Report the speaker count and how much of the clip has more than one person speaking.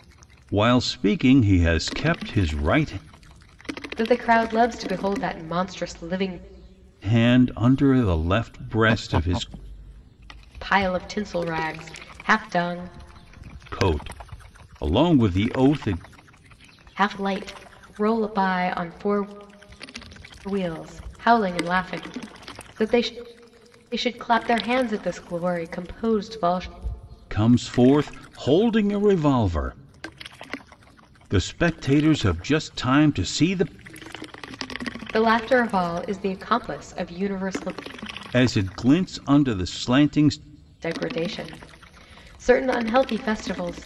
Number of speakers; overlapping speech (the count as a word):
two, no overlap